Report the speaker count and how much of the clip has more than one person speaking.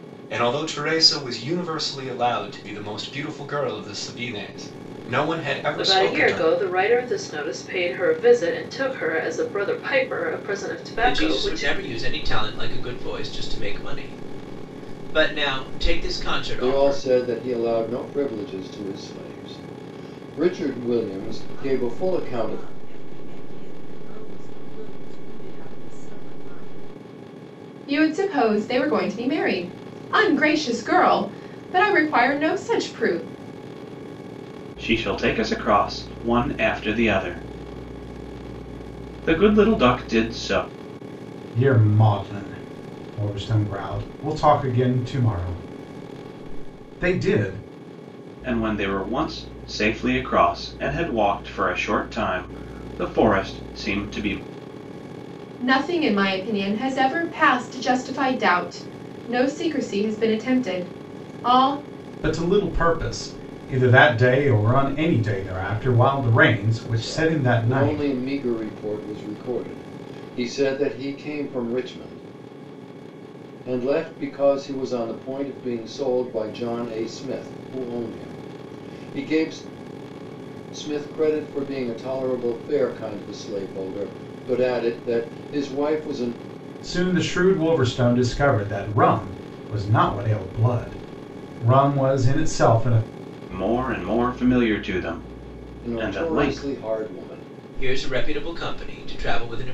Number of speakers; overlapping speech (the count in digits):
8, about 6%